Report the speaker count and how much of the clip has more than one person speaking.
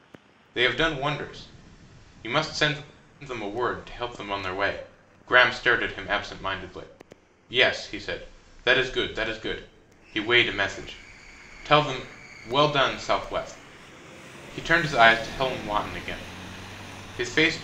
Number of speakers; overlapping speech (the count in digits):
1, no overlap